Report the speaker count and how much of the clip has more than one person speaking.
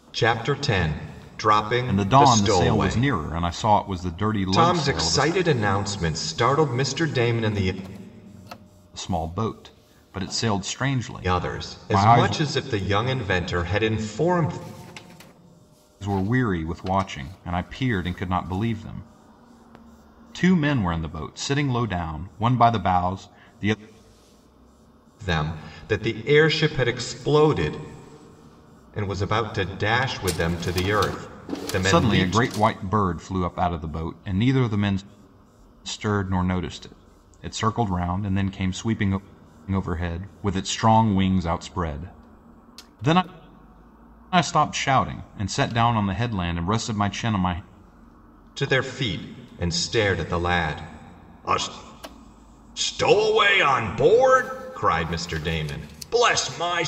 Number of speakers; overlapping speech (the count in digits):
2, about 7%